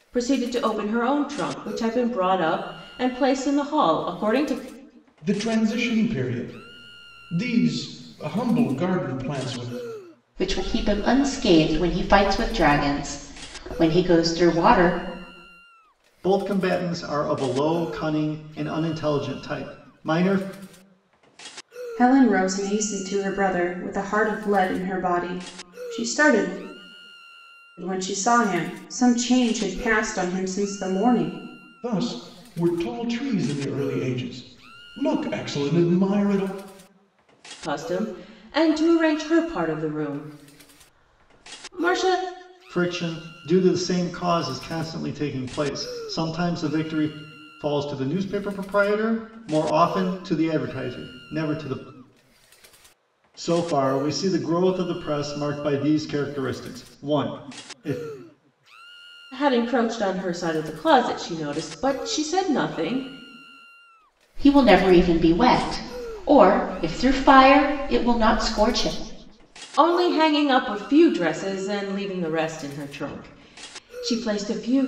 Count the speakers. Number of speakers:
5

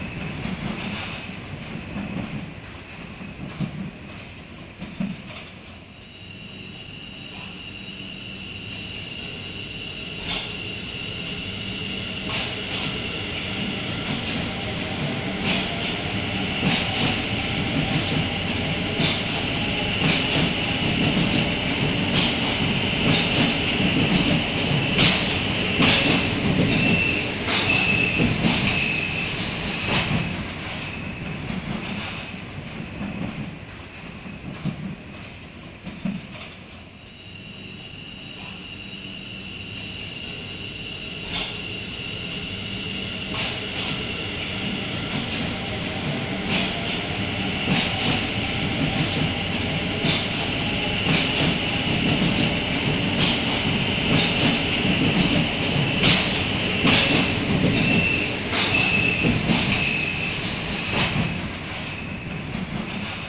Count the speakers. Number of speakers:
0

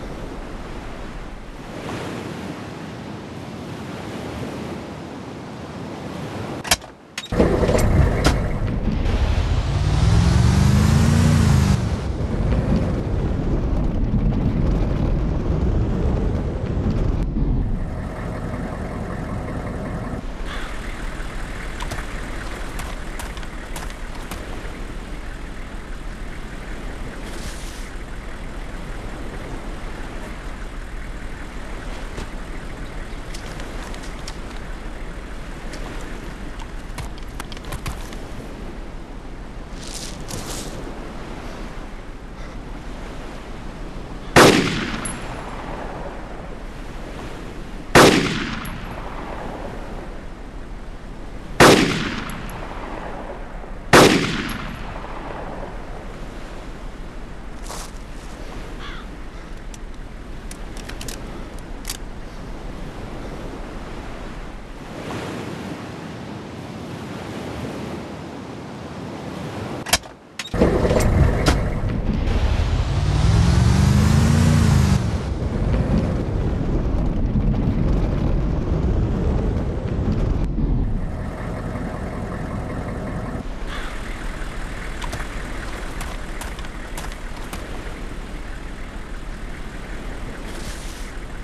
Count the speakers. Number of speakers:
0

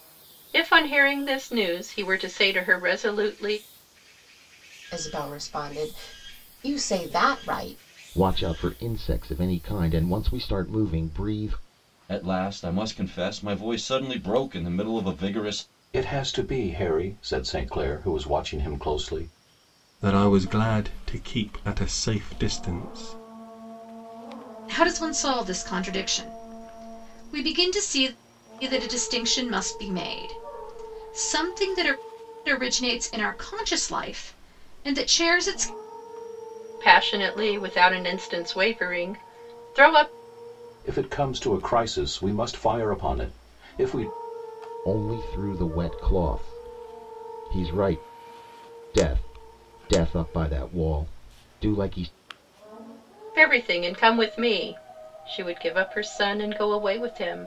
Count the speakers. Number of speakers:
7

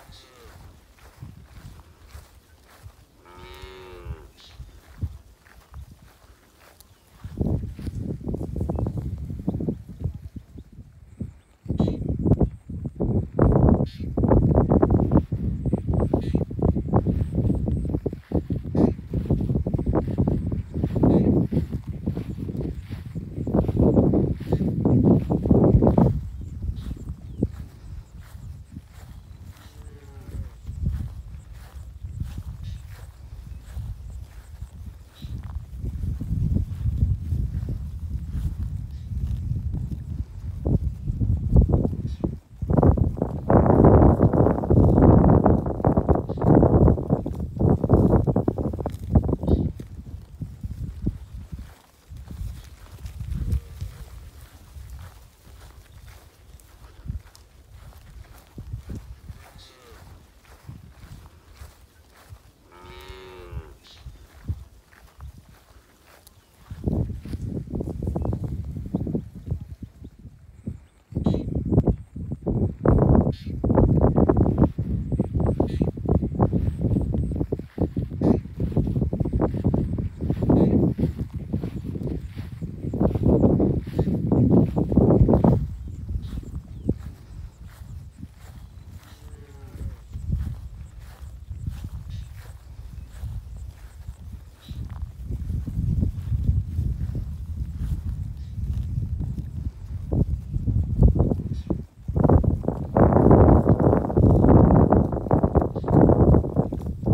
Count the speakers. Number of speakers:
0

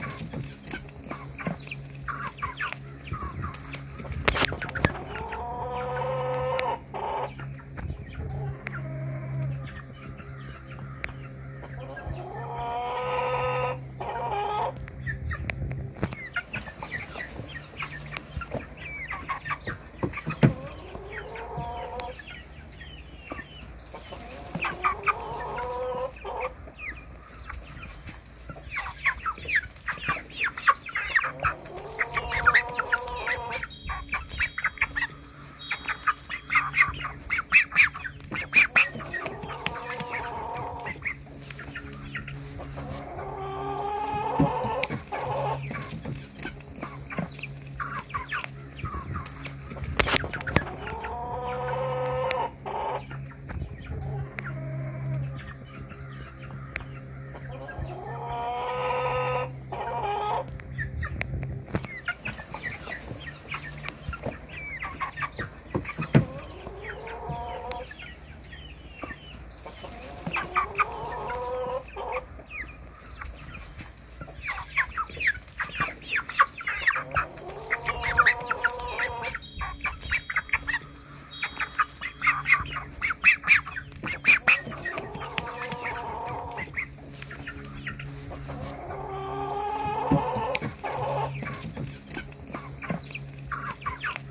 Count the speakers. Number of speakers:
0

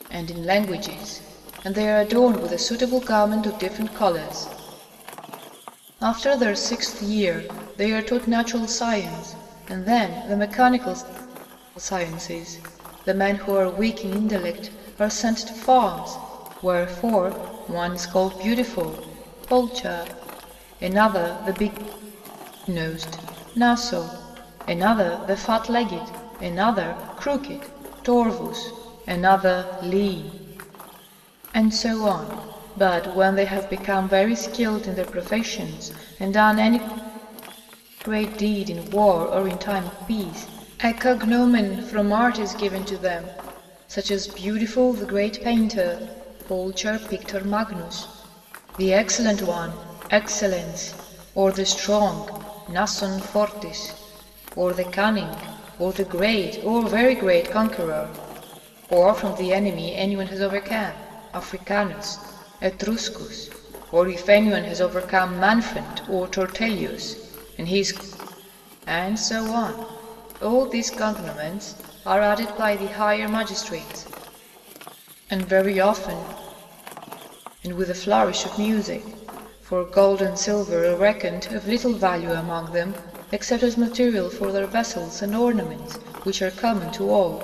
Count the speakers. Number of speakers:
1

